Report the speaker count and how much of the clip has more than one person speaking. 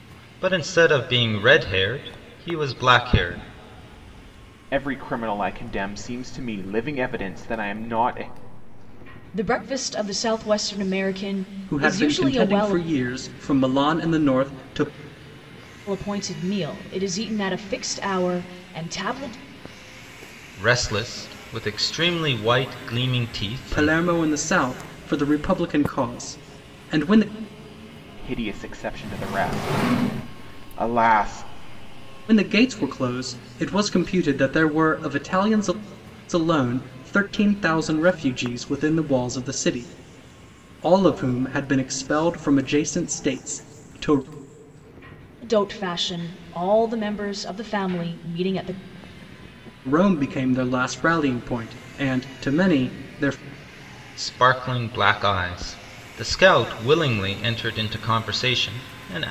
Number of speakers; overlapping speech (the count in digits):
4, about 3%